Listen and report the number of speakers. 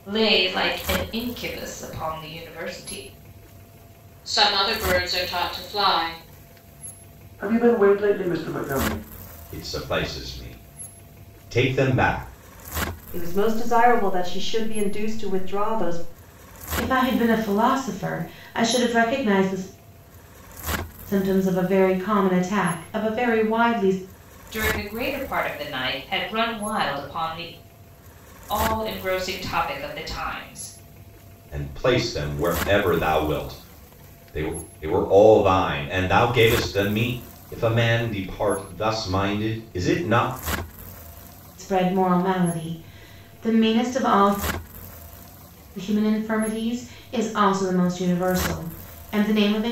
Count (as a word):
six